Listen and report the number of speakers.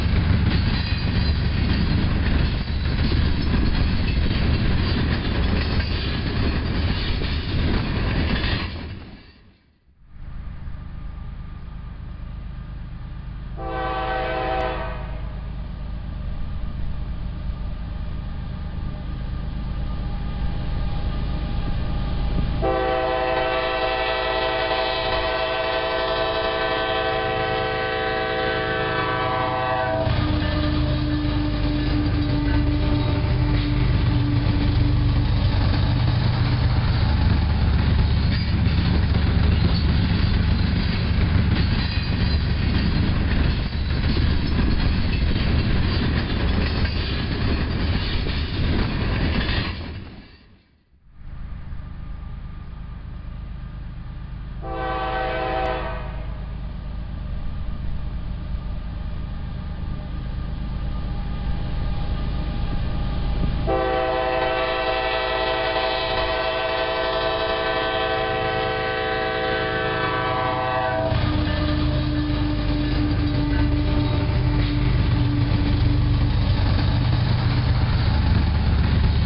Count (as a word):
zero